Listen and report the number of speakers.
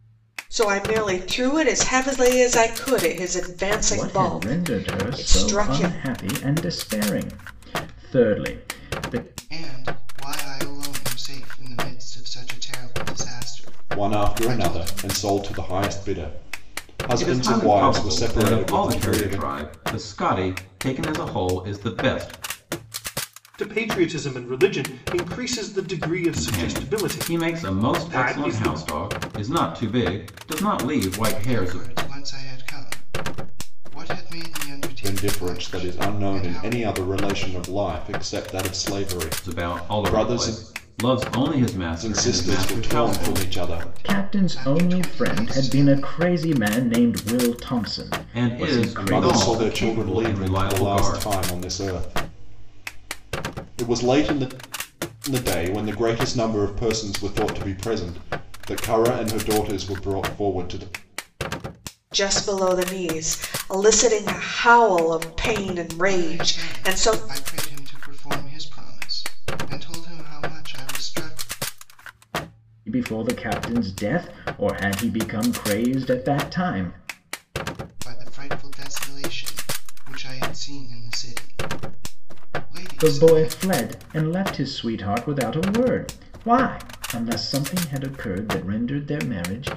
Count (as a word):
six